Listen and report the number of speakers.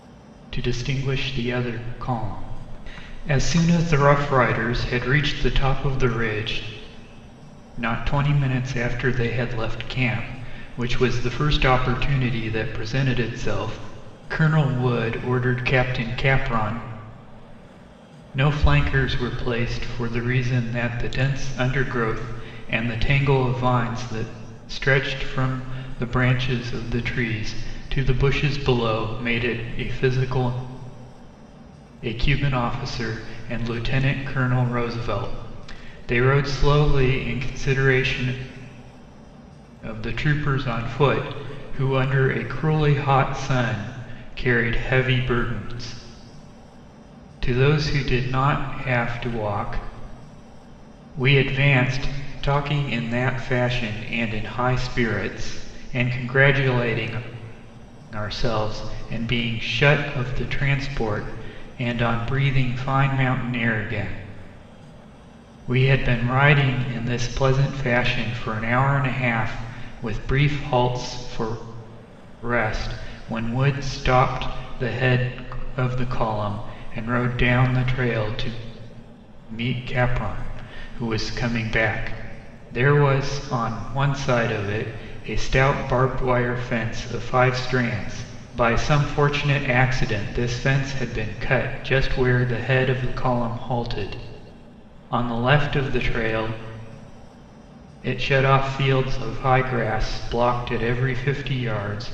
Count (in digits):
1